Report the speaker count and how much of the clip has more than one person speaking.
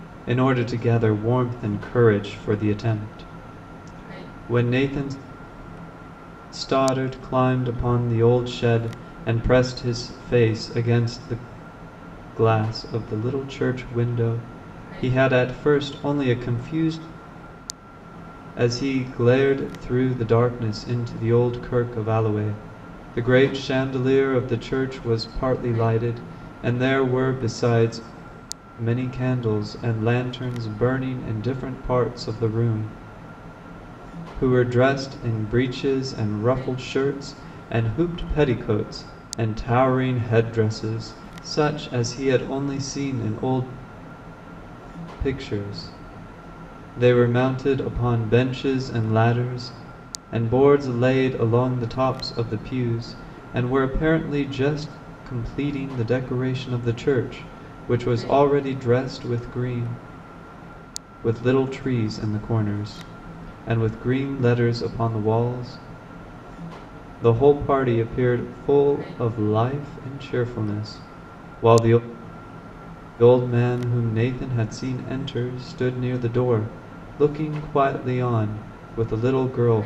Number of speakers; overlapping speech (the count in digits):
1, no overlap